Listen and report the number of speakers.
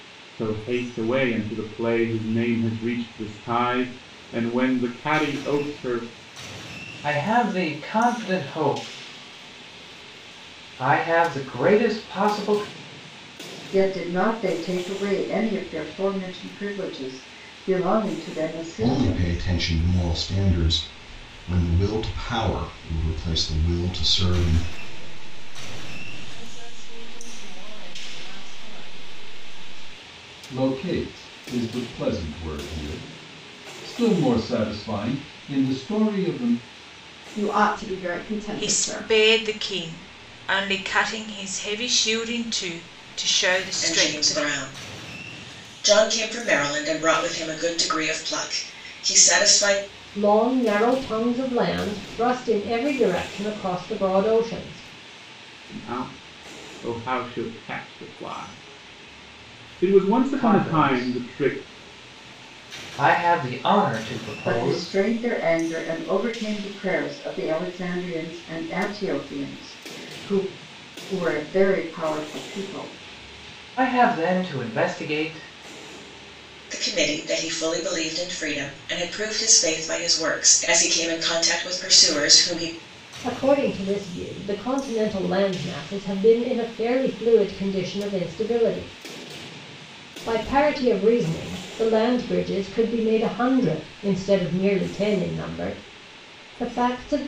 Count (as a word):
ten